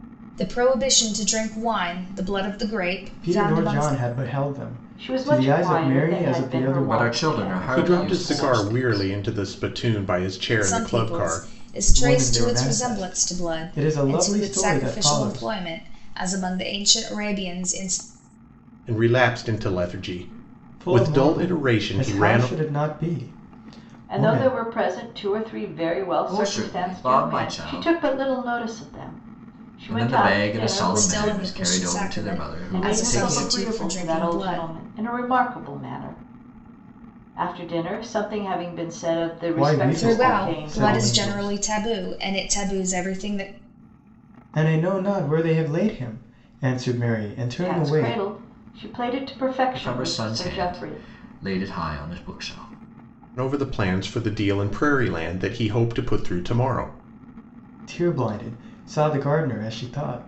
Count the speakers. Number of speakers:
5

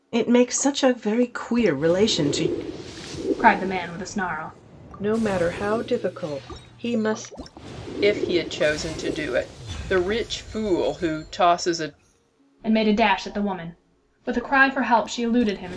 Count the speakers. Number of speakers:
4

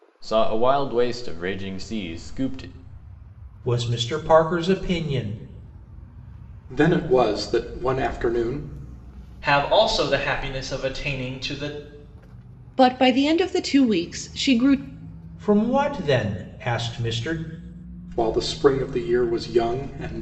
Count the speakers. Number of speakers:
5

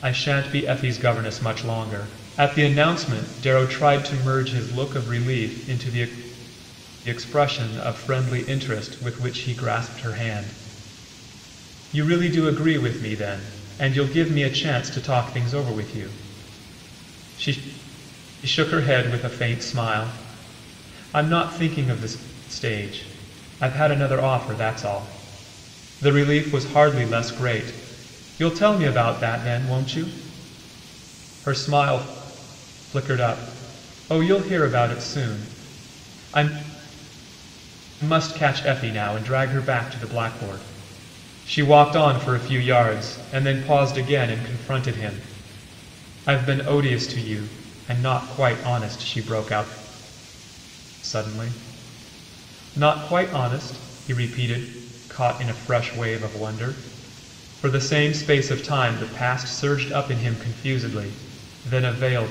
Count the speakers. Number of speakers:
1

